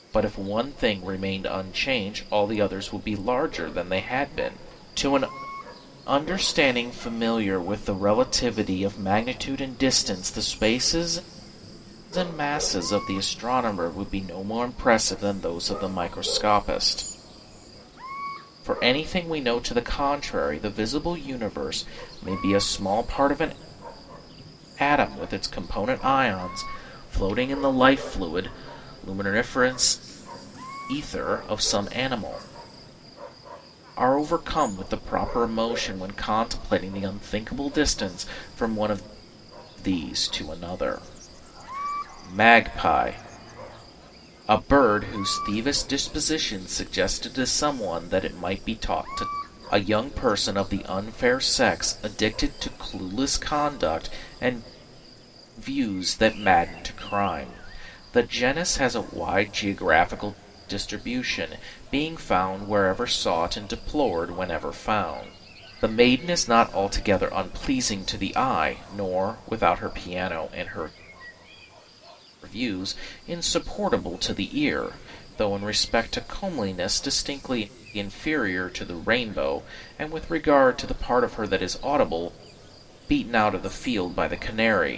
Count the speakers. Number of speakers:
1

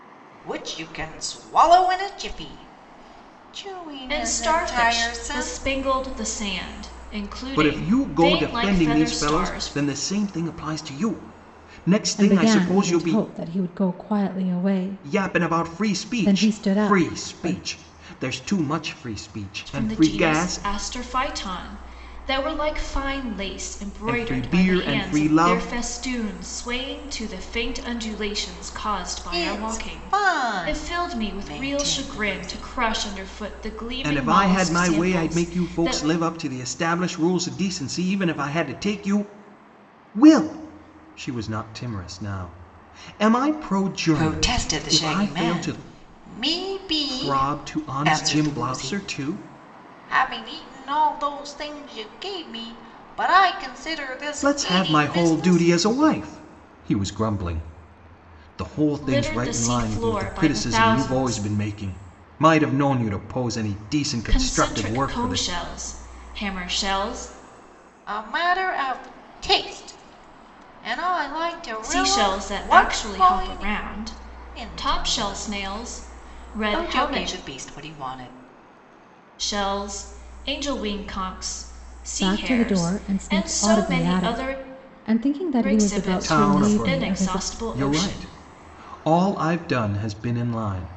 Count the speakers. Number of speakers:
4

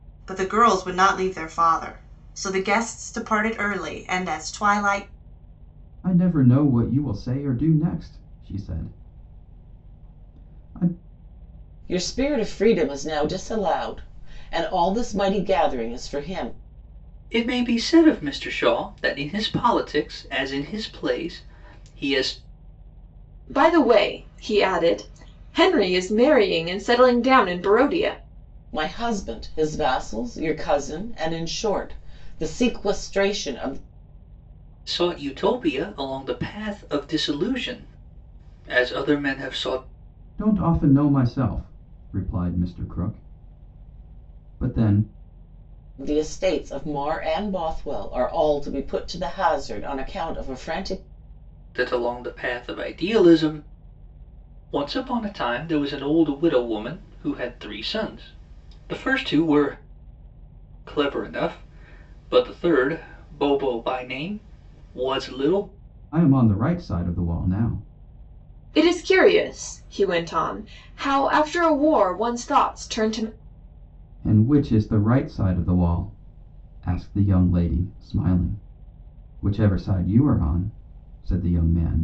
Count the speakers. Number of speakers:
5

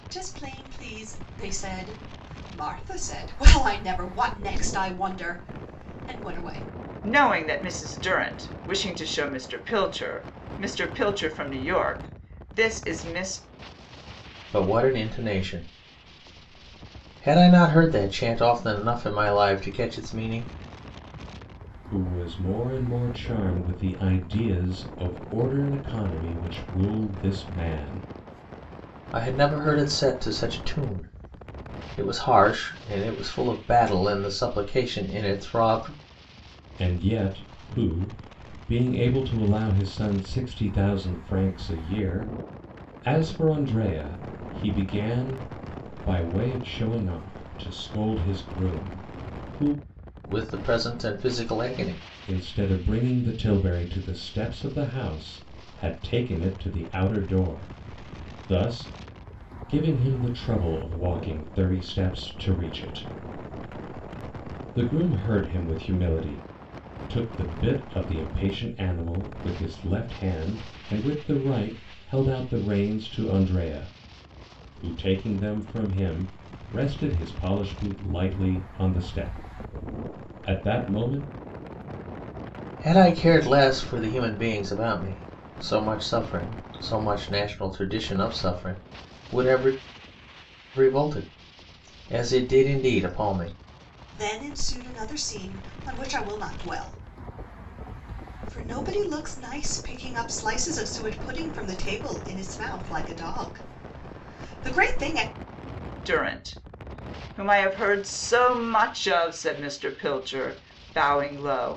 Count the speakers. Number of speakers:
4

